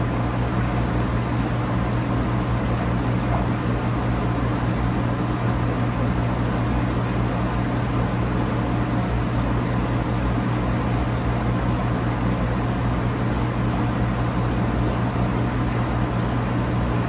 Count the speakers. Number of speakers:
0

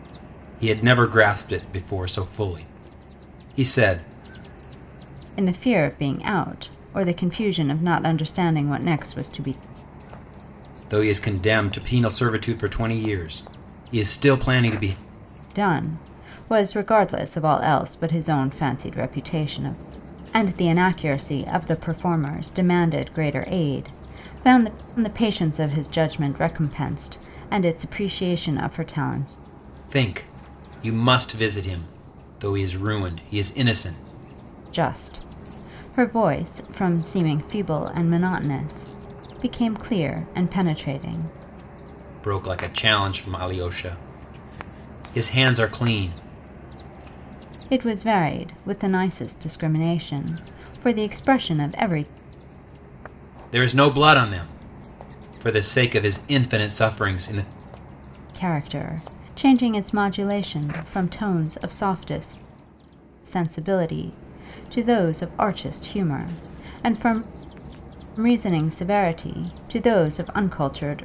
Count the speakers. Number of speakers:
2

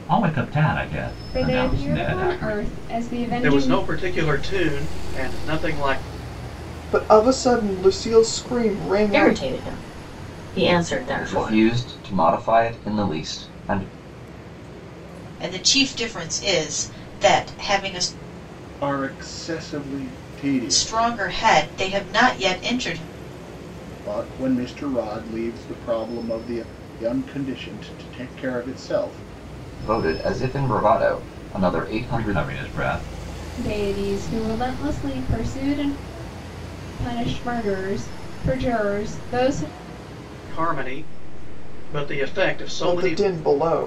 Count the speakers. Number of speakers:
8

